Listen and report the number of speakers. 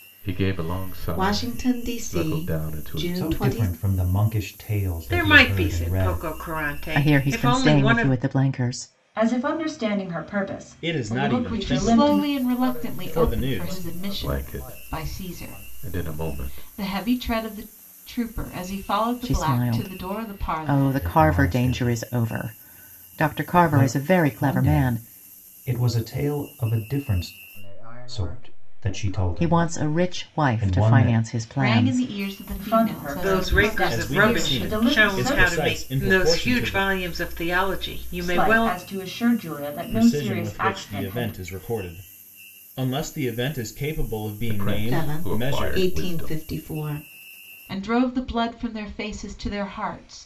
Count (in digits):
9